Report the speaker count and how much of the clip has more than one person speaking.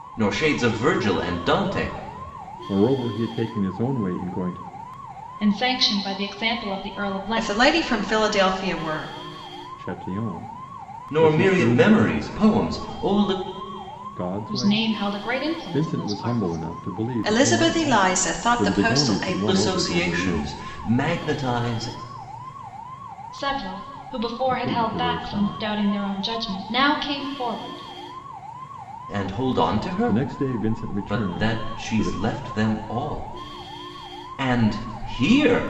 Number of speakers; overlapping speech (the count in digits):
4, about 26%